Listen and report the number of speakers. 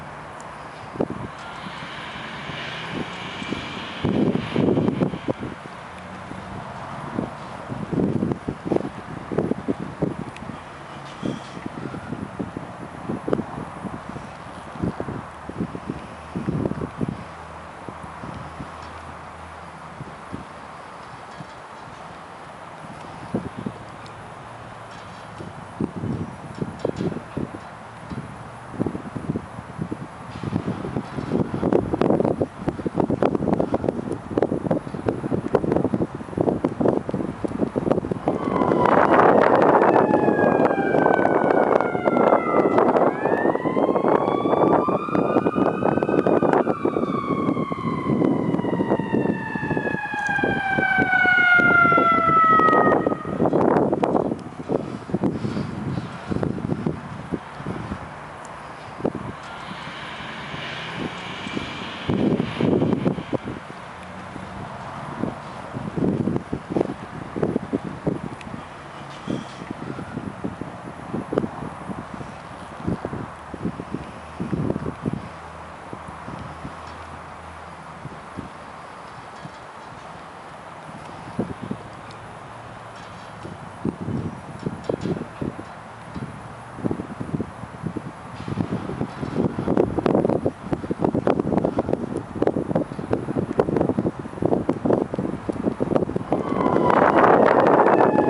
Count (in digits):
0